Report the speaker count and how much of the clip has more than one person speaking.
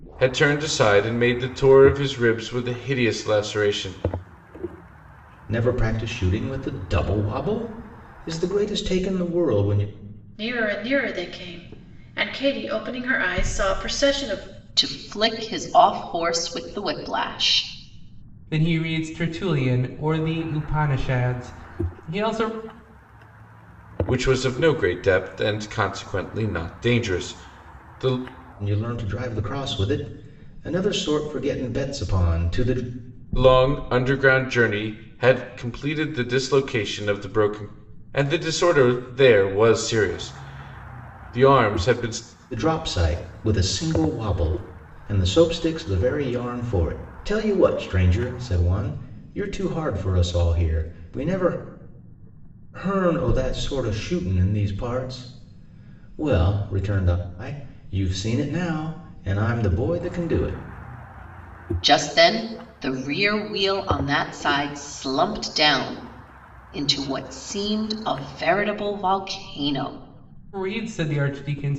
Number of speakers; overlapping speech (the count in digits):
5, no overlap